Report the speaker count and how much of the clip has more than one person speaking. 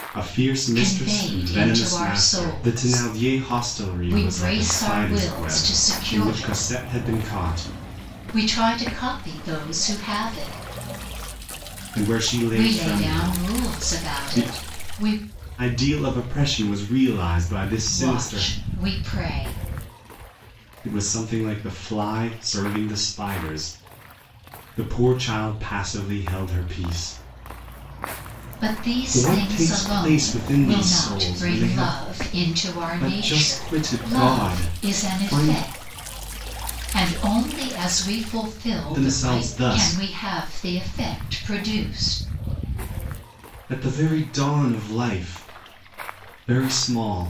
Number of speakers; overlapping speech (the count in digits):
2, about 29%